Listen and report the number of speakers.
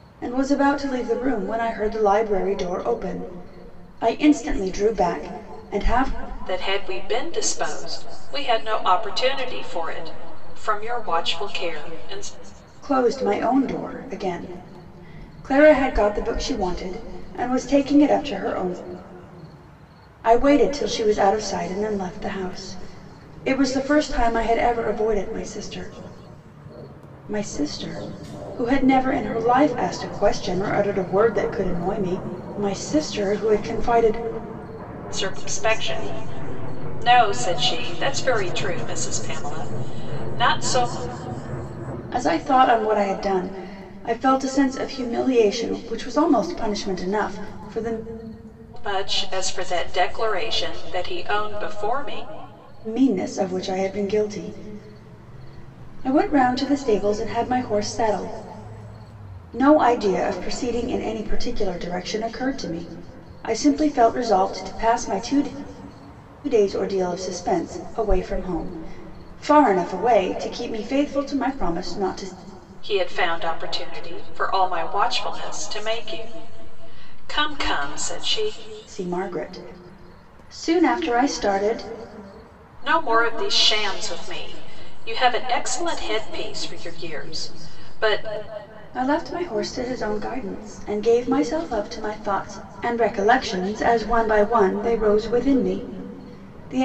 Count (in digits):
2